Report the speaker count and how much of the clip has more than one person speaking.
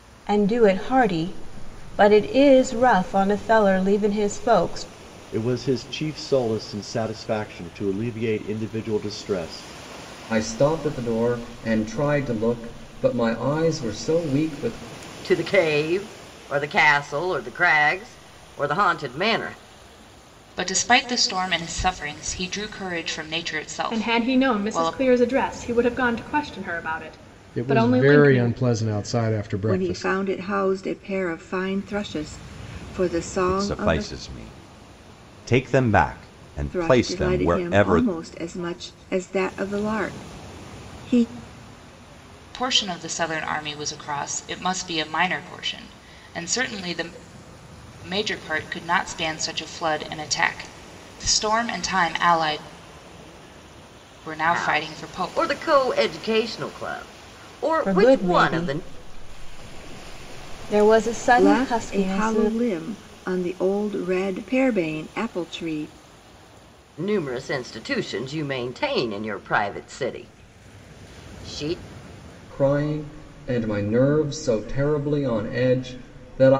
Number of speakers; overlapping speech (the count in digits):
9, about 11%